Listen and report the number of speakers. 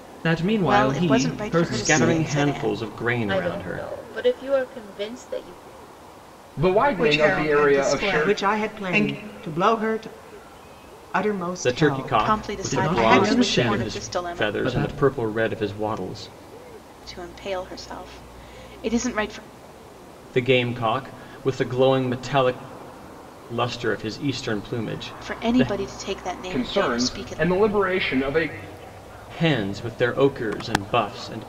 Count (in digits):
7